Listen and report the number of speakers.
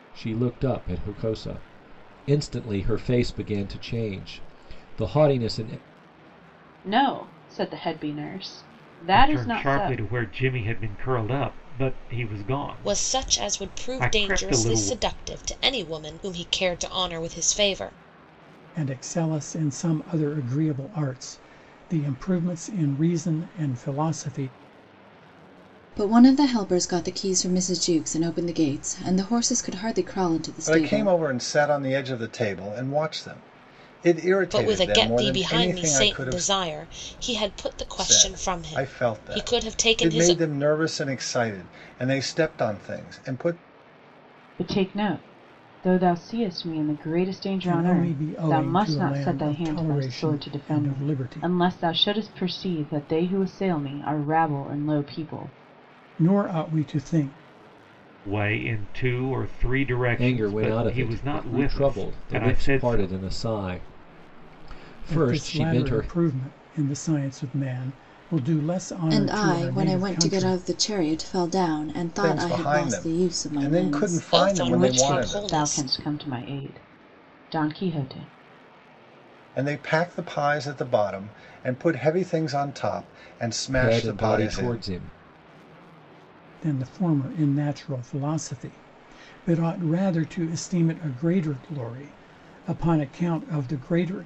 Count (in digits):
7